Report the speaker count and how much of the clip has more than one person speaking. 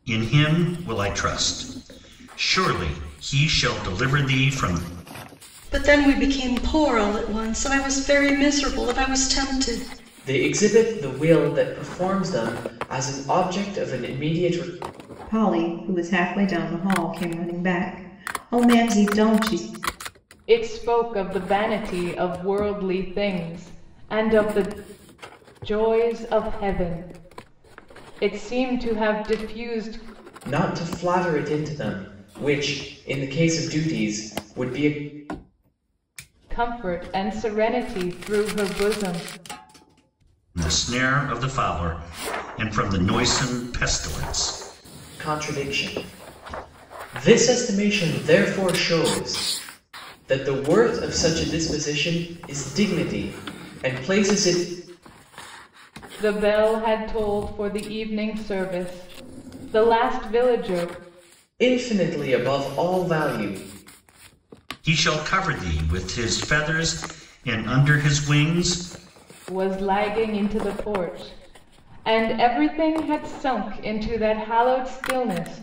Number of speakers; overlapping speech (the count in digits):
5, no overlap